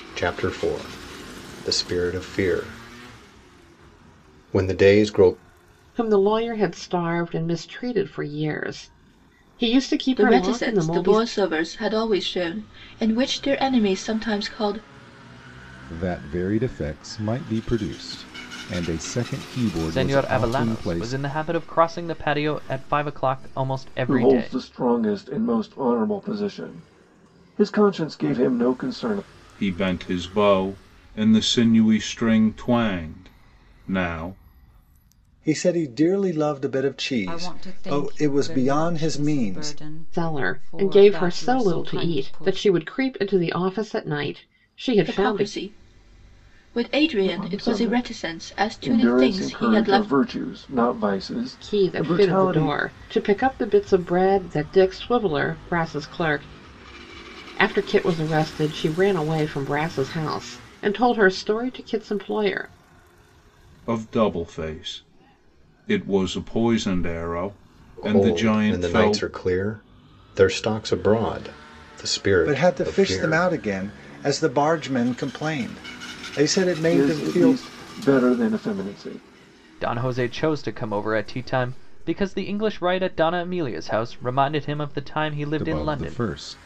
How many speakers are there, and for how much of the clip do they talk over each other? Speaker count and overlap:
nine, about 19%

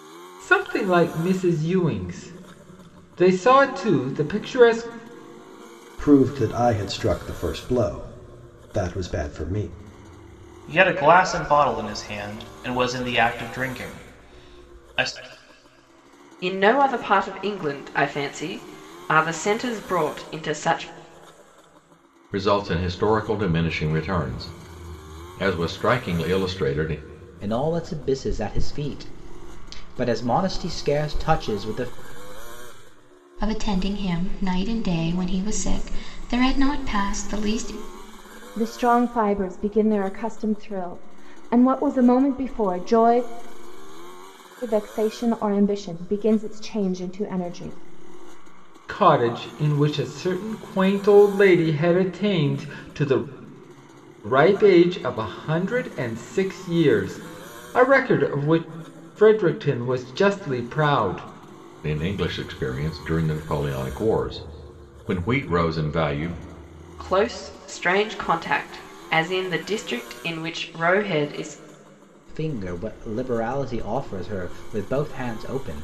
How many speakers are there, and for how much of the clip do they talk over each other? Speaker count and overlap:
eight, no overlap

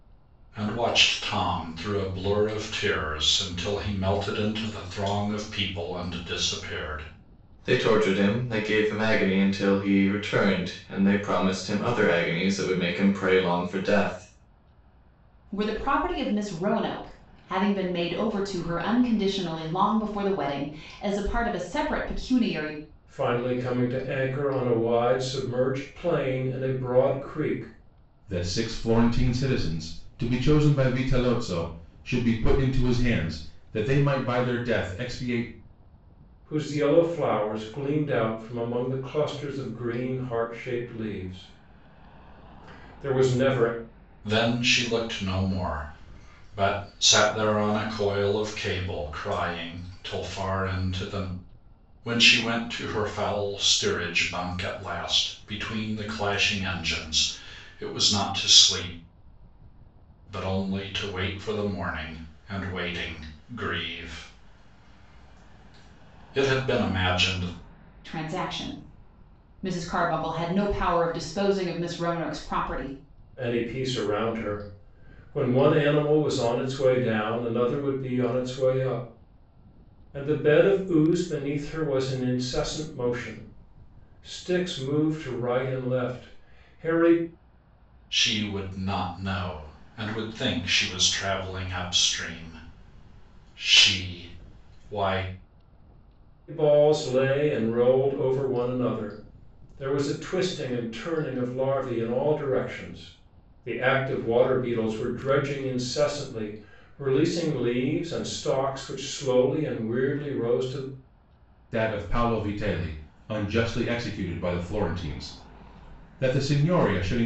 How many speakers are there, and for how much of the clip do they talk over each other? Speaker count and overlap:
five, no overlap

